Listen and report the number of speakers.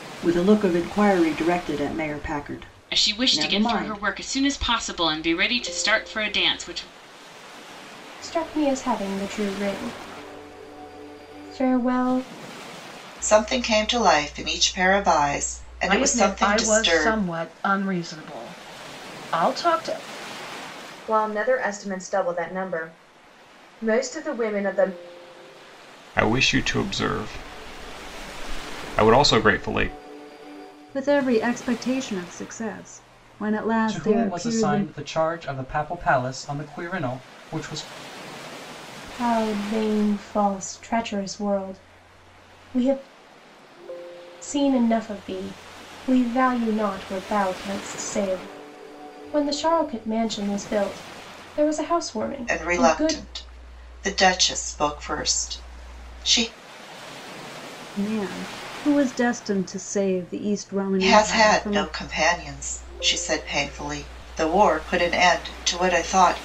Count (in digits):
9